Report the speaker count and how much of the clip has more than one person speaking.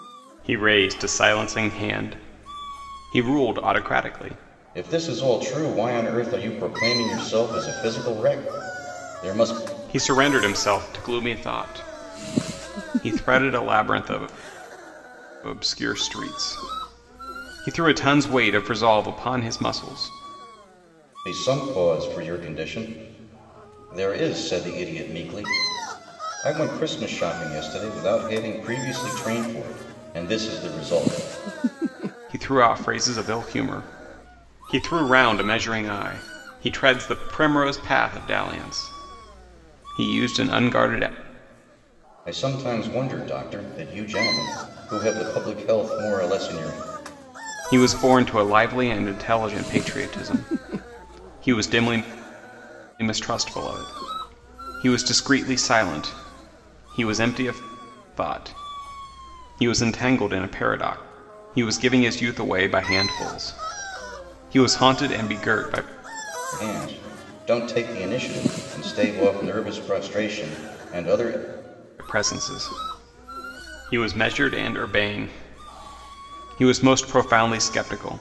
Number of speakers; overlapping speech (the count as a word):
two, no overlap